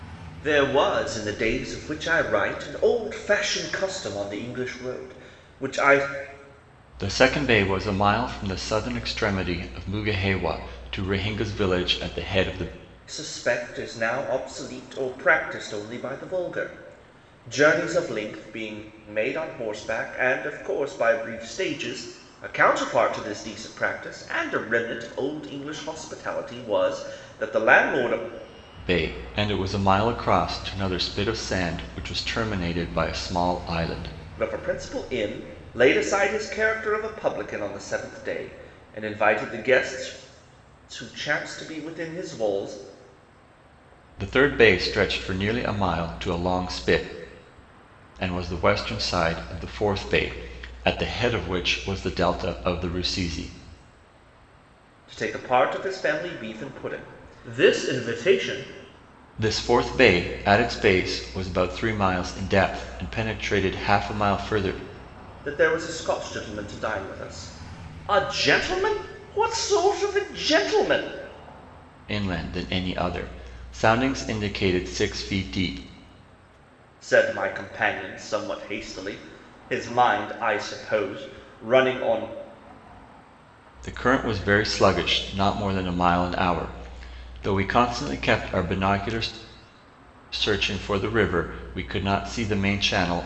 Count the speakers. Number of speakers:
2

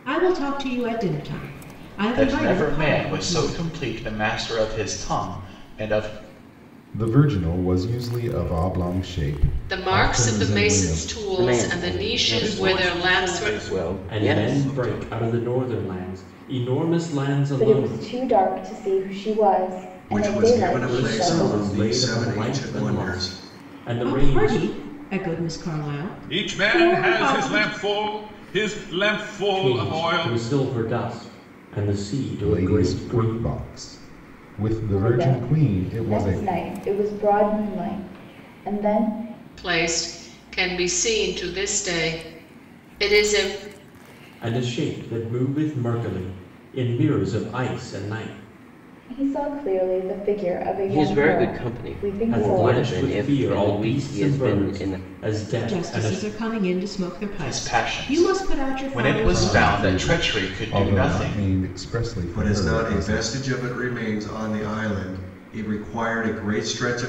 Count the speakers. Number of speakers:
9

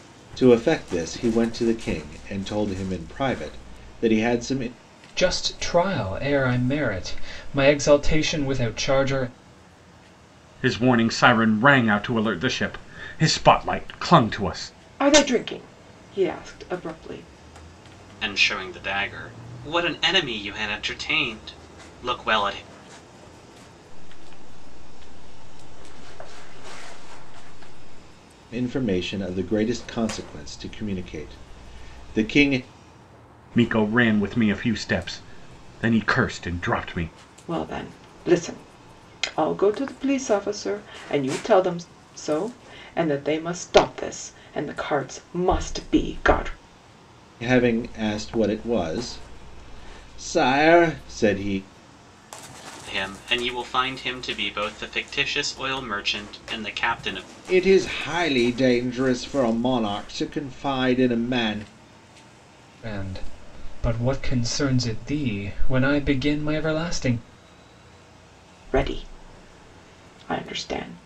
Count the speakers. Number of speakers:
6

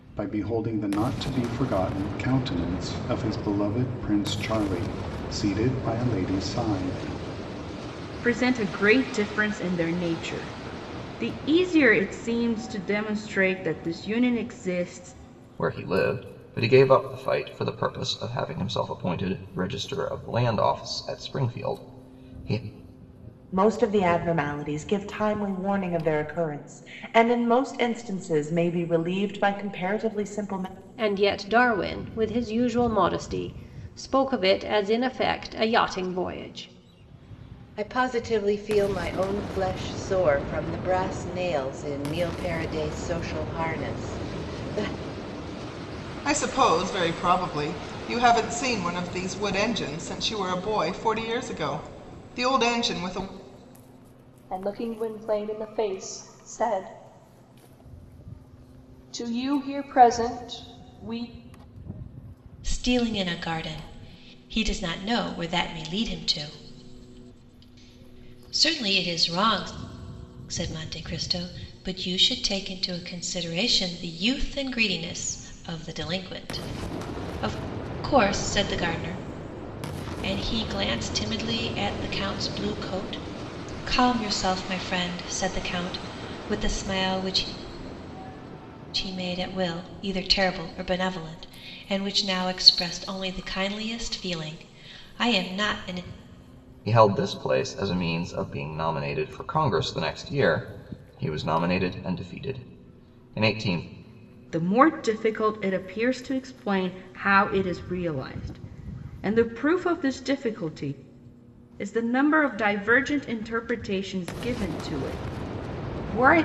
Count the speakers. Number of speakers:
9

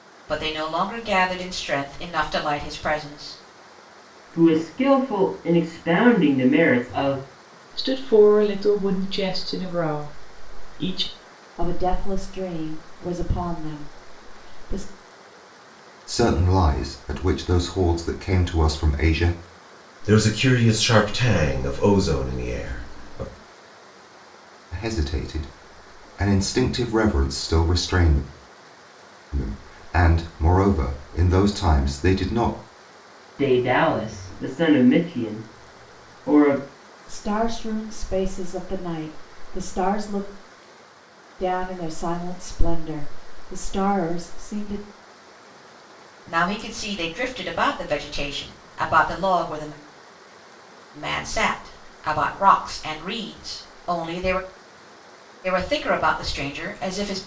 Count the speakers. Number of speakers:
6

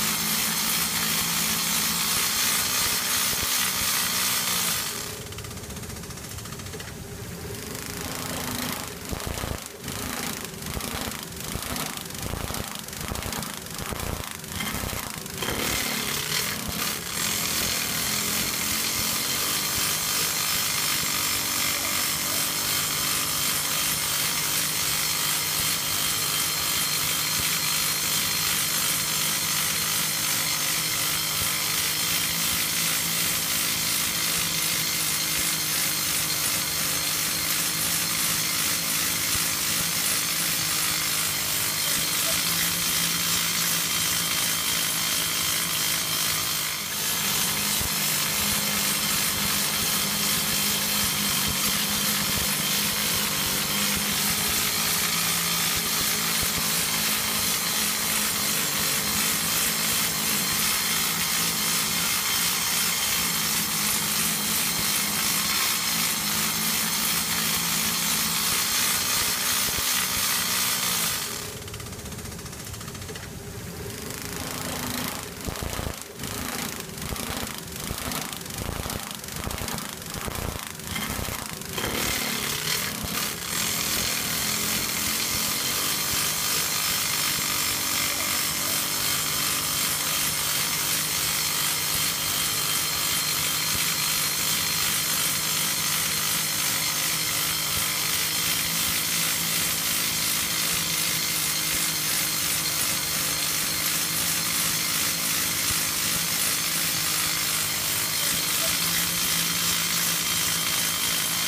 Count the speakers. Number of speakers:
0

